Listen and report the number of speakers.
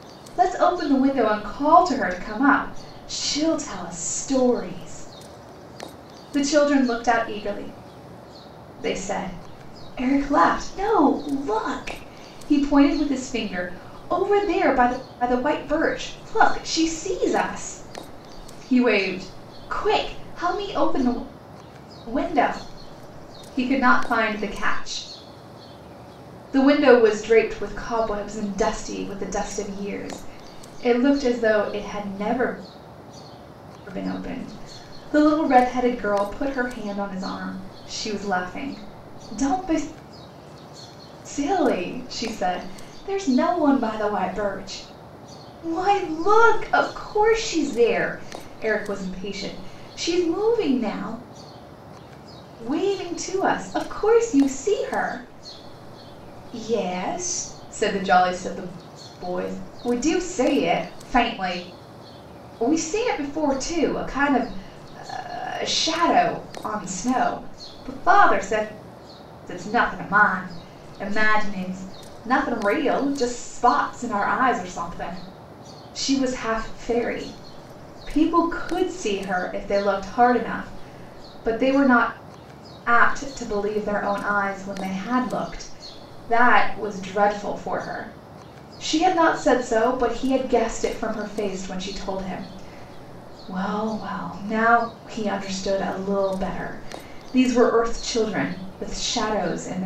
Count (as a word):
one